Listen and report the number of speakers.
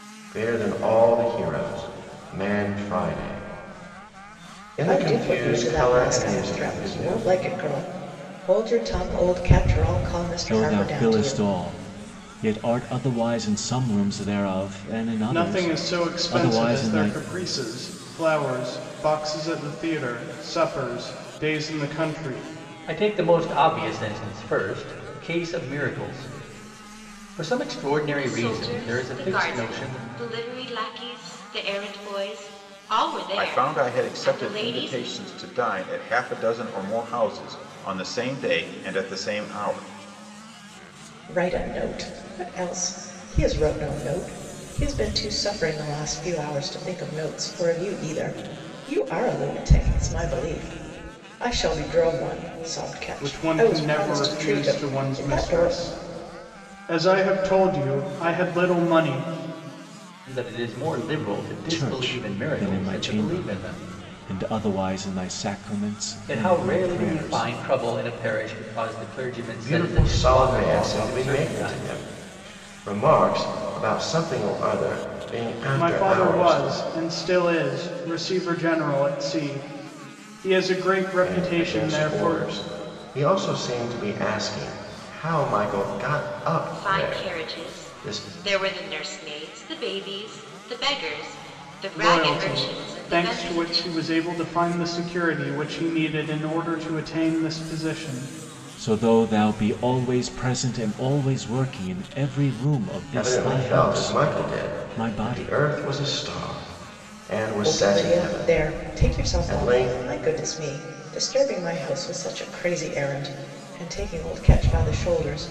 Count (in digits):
7